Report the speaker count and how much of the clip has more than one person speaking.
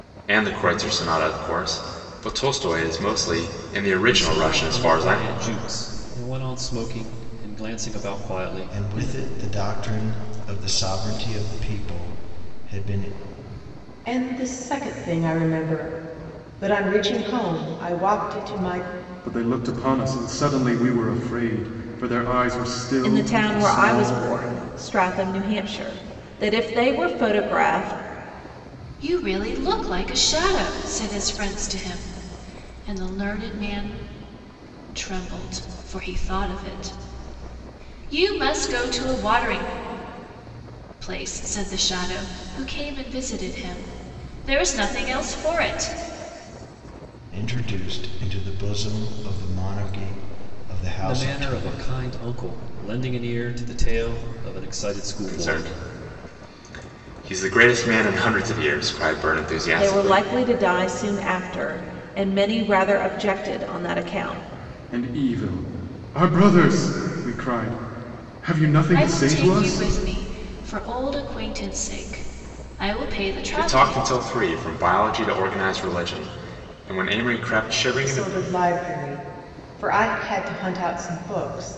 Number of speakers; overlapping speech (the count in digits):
7, about 8%